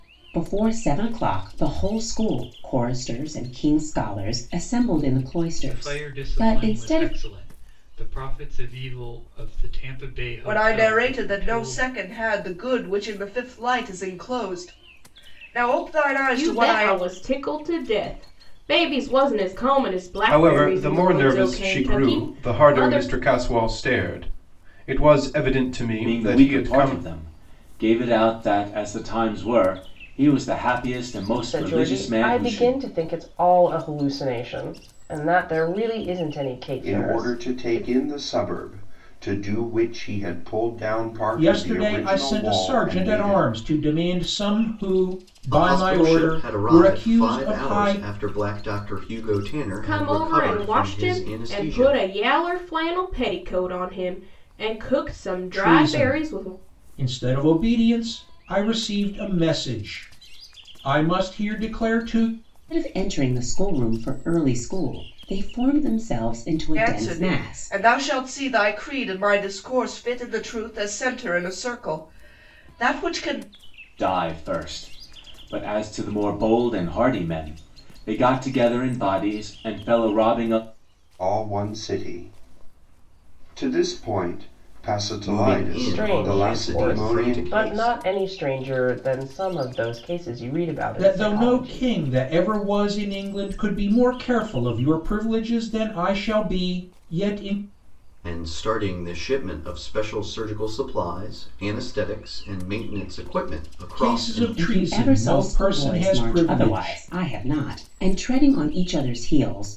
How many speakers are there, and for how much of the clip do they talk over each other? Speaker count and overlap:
10, about 24%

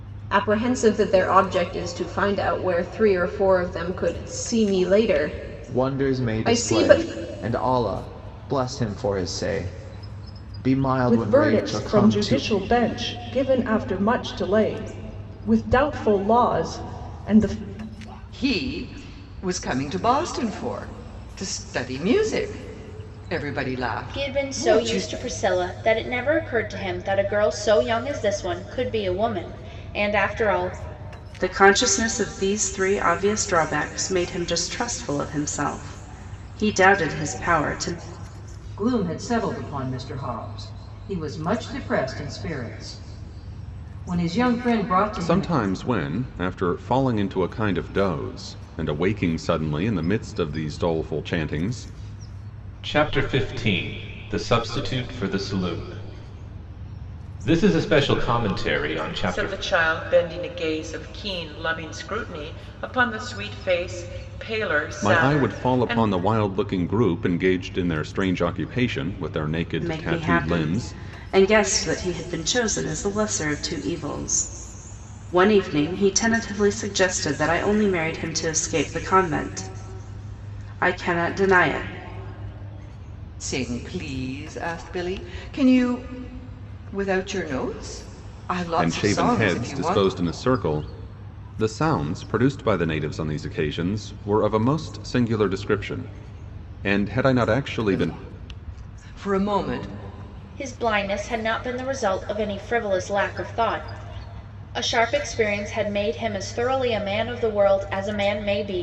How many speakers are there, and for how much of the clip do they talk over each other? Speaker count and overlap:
10, about 8%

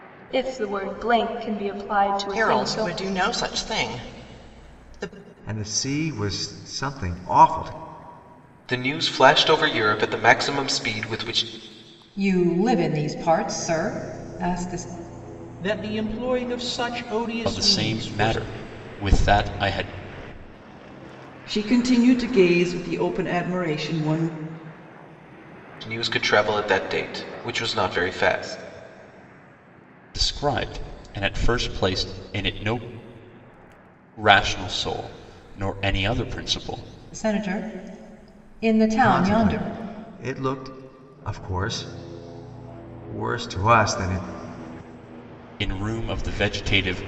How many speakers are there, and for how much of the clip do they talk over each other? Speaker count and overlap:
8, about 5%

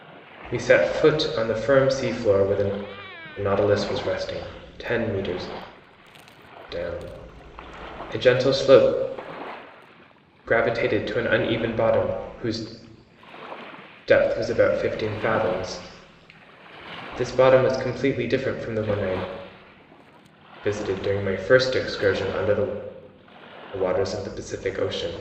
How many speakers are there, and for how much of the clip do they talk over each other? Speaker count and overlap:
1, no overlap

